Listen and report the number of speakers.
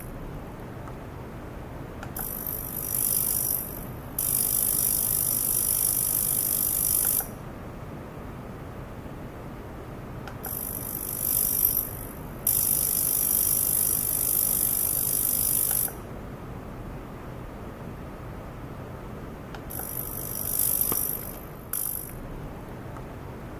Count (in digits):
0